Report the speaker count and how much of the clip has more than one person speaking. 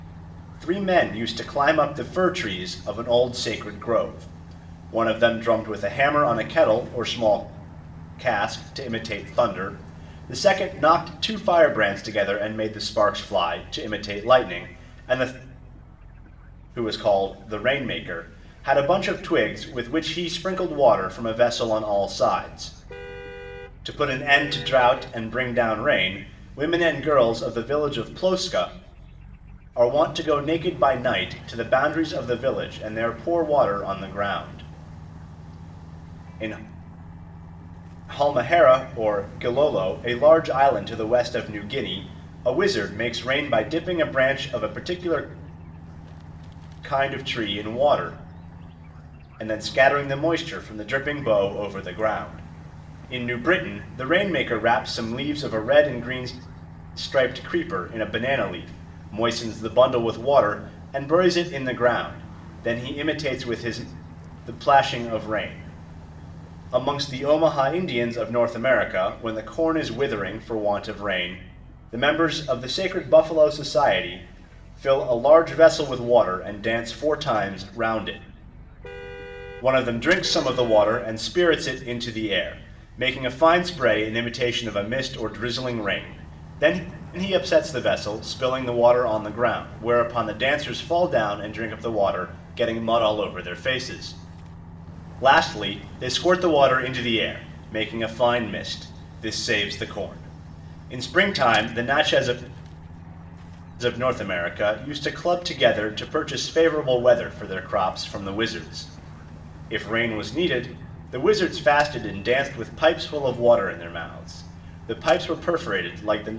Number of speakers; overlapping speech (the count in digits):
1, no overlap